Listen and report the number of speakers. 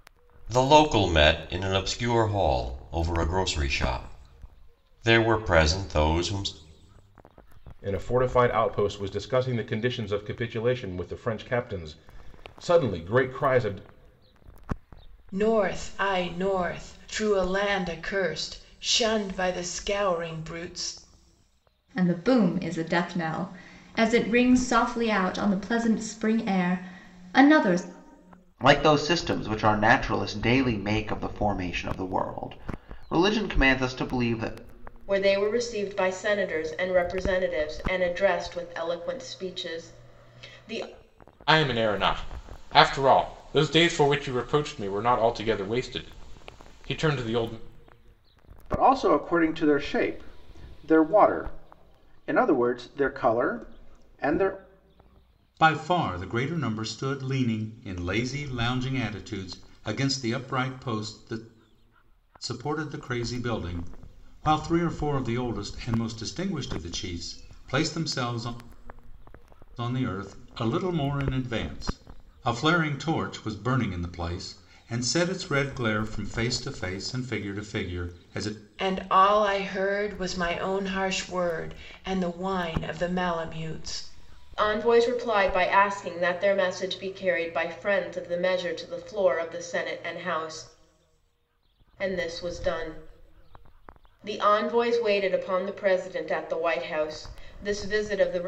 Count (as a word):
nine